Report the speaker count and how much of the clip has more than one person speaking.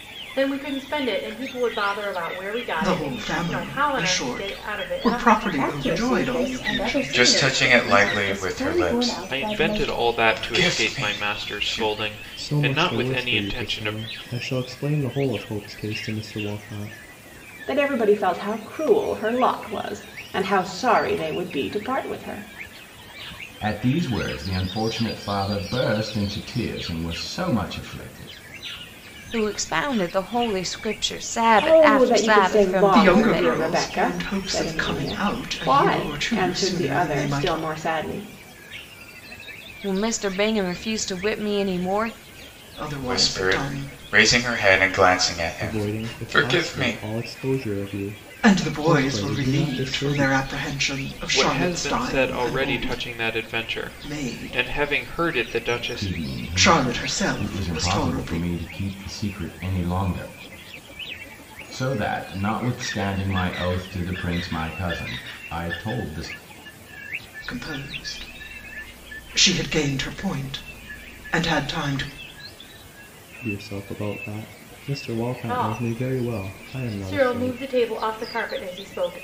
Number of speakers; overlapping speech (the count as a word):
nine, about 36%